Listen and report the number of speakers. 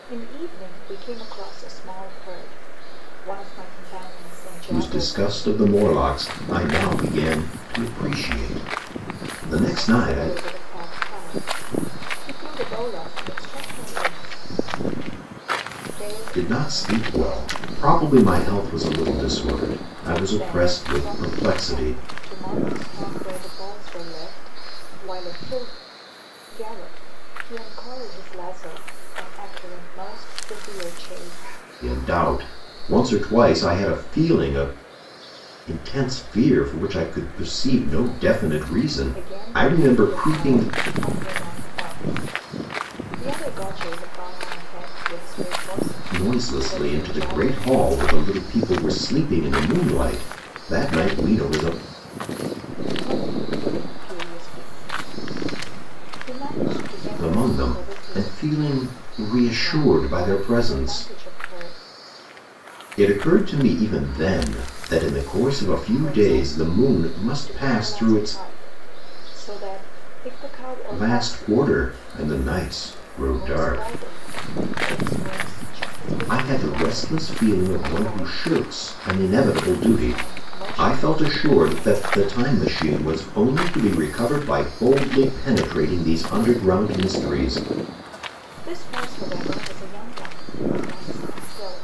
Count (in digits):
2